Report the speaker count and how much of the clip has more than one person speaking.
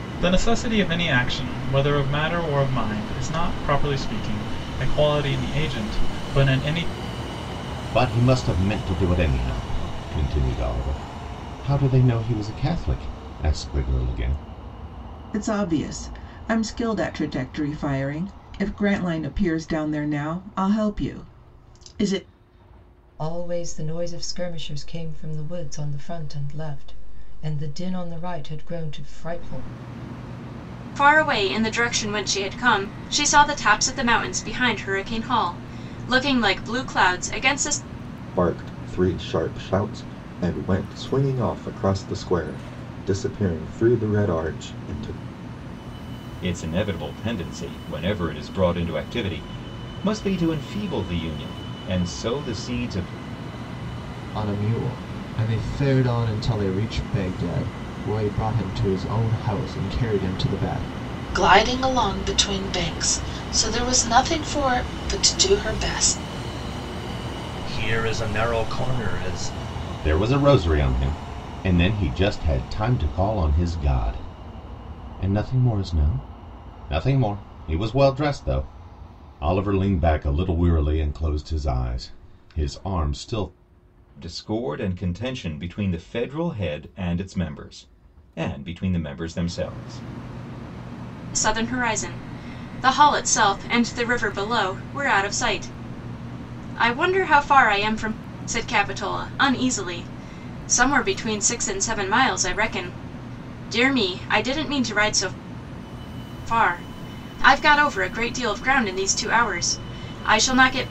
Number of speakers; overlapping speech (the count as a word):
ten, no overlap